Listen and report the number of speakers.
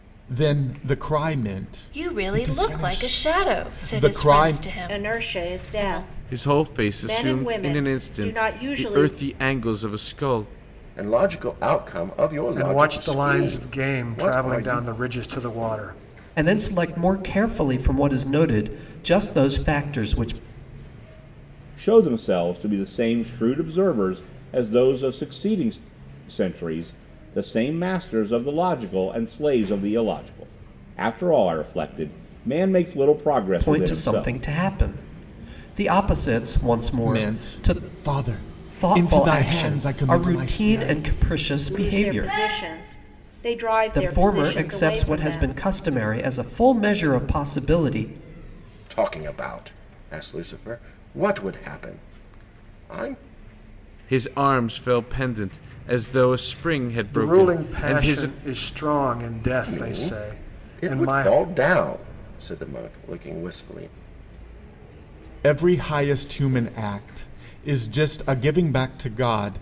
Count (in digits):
8